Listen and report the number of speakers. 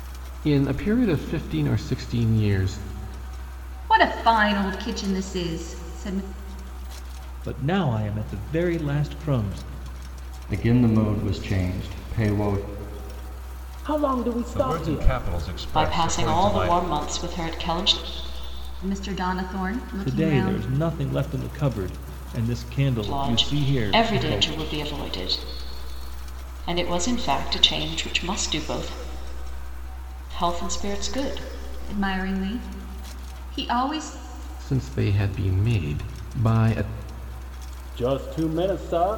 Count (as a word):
seven